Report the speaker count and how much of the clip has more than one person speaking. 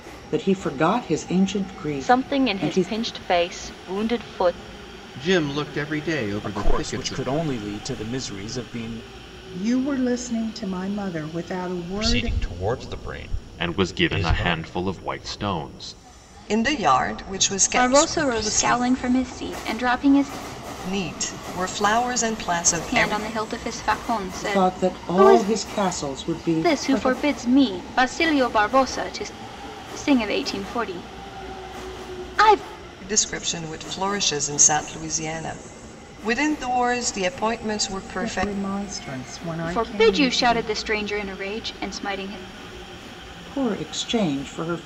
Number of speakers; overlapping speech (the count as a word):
nine, about 18%